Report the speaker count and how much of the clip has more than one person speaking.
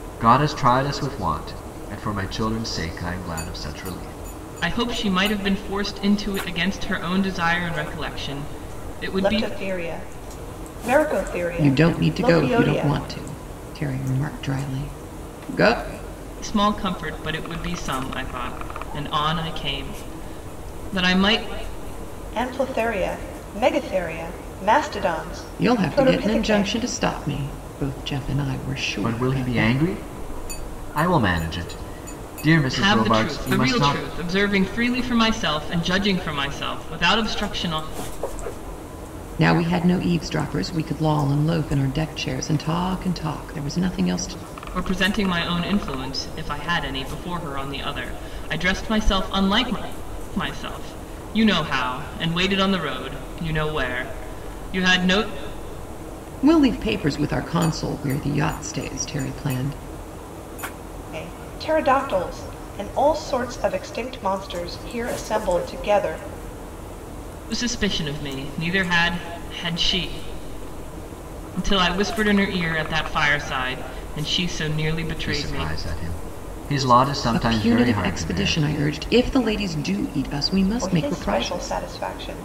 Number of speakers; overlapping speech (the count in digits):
4, about 10%